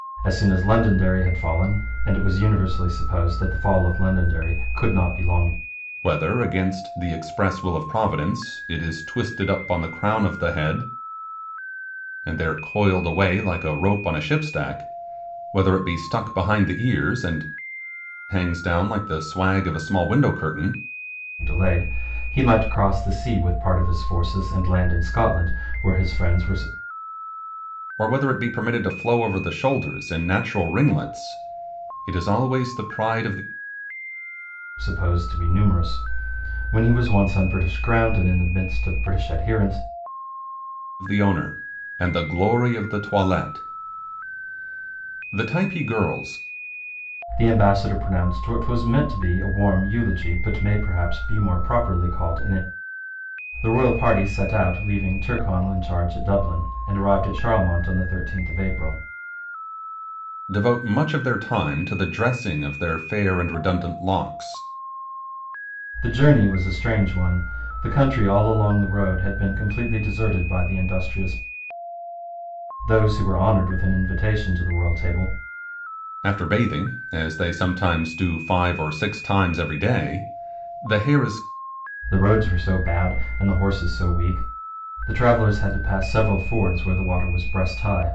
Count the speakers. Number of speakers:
two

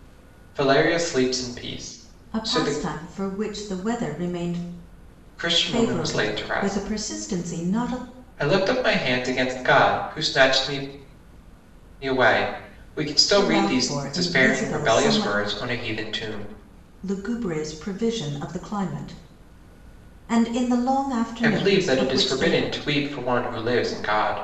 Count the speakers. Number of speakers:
two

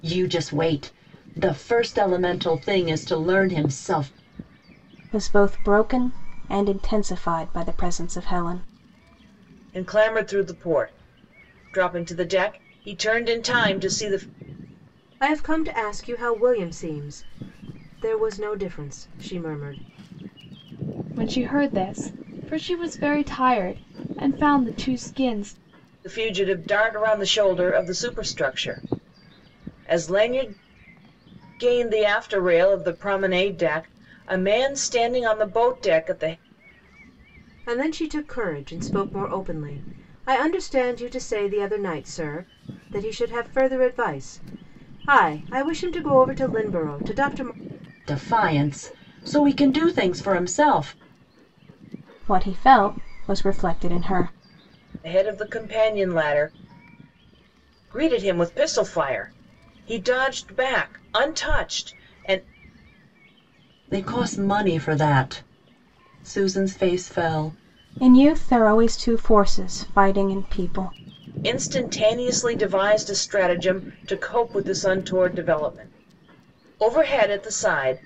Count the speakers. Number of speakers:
five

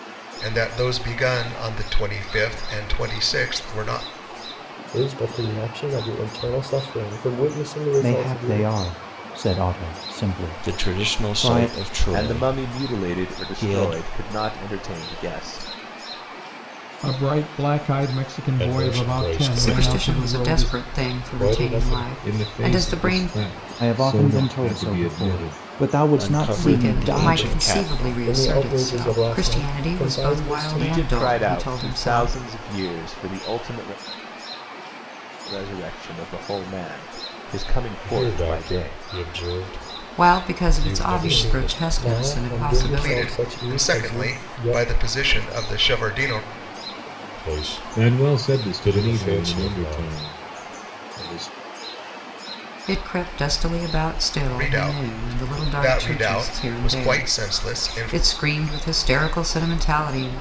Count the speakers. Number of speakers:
nine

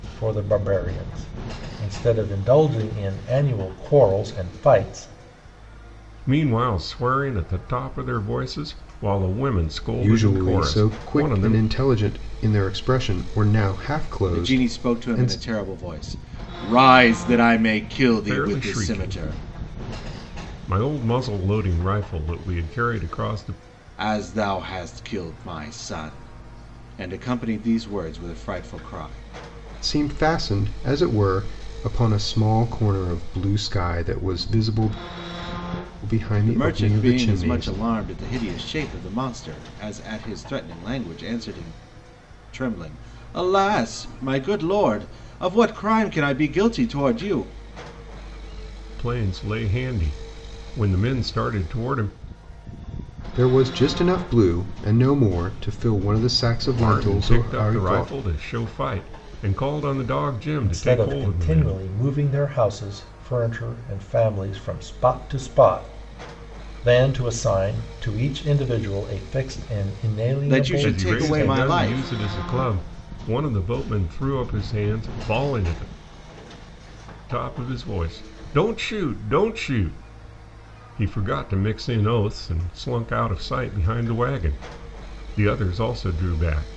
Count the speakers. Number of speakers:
four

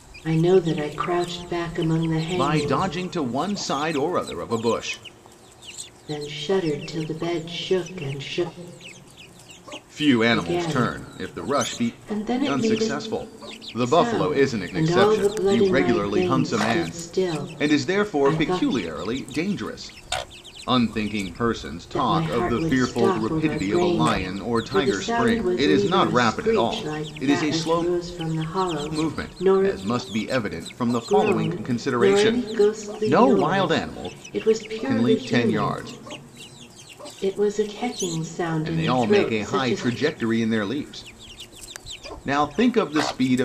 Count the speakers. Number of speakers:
two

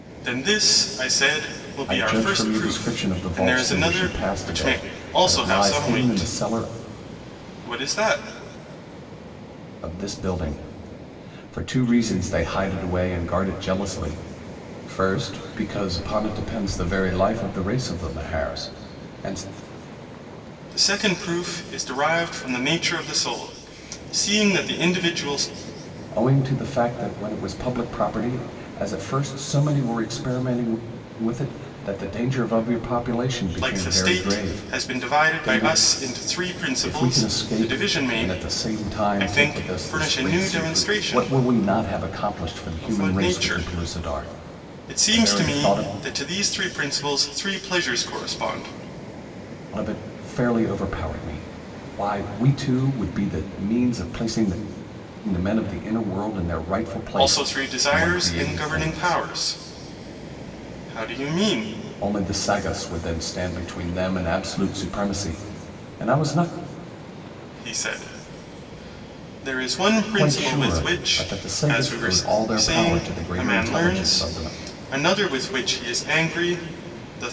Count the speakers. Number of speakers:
two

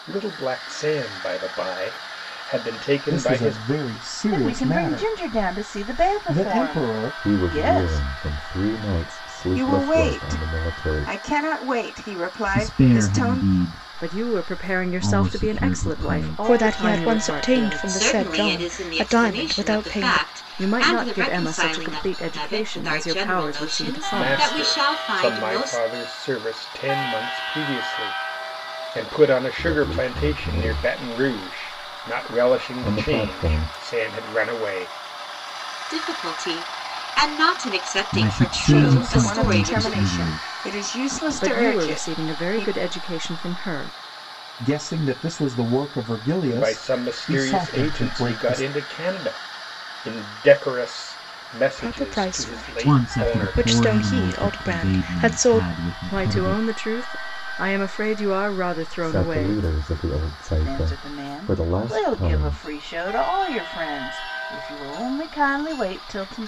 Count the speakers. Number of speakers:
nine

